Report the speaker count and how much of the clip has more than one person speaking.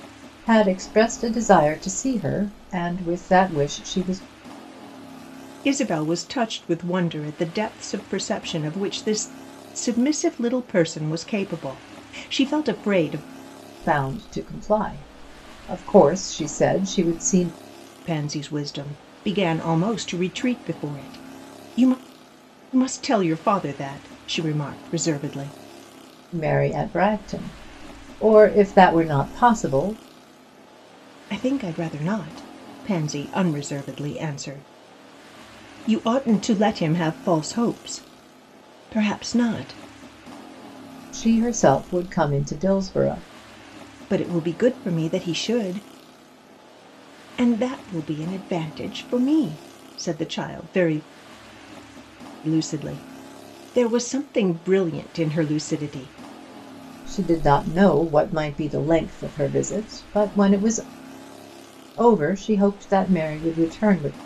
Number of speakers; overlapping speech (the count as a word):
two, no overlap